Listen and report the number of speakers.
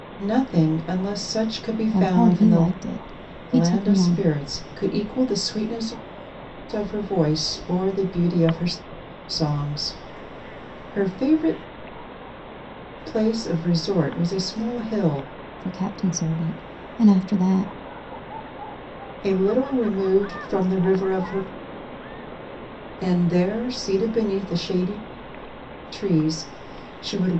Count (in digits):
2